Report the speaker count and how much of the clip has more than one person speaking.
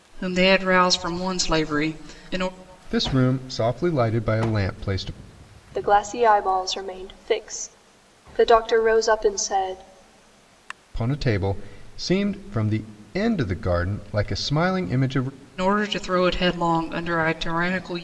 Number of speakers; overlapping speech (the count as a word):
three, no overlap